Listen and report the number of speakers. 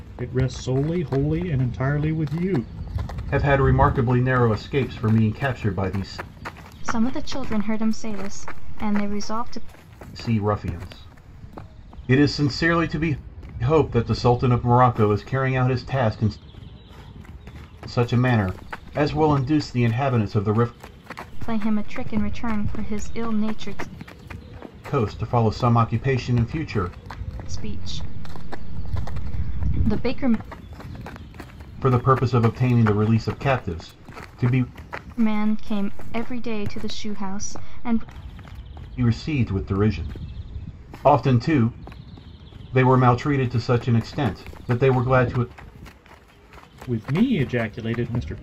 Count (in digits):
3